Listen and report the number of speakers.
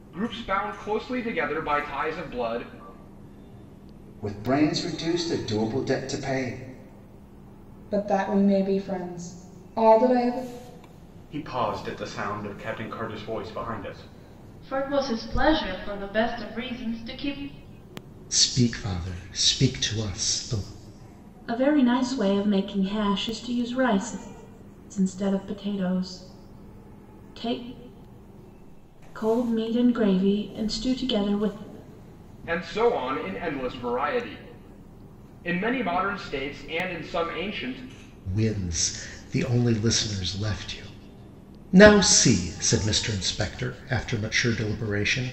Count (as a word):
seven